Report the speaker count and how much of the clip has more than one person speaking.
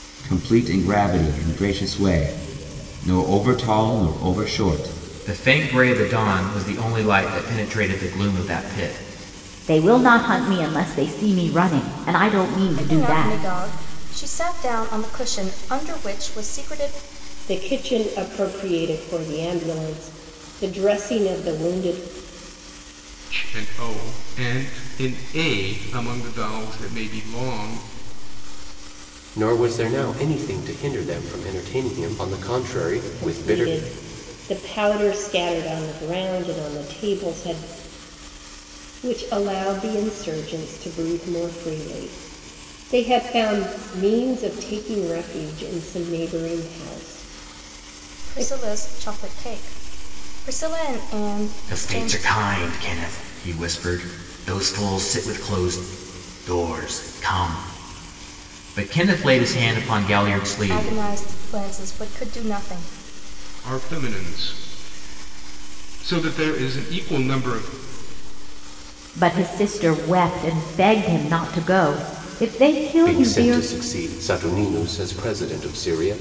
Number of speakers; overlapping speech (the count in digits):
7, about 5%